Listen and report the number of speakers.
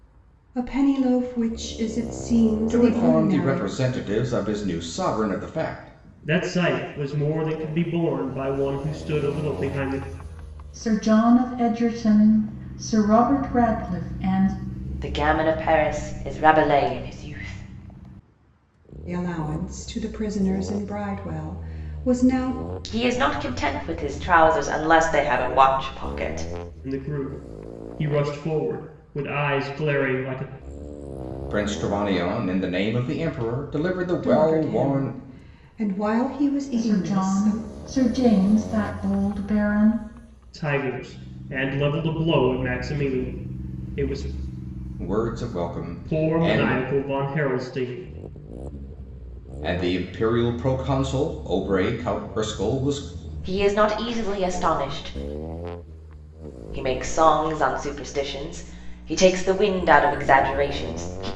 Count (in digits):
5